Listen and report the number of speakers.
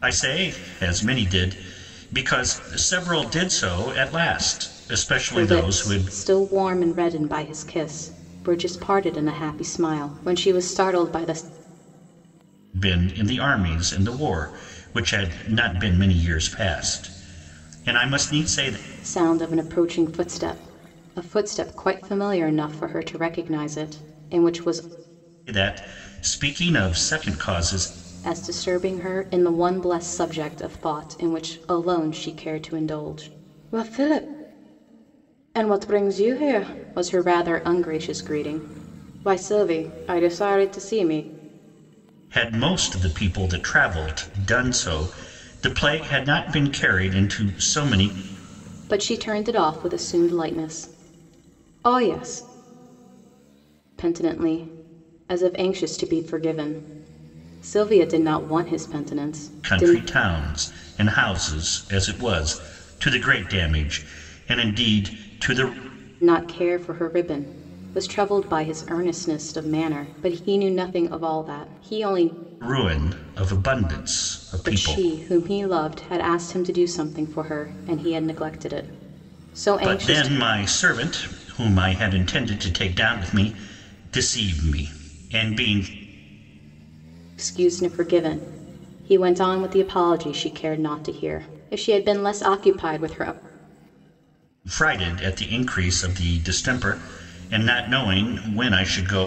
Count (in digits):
2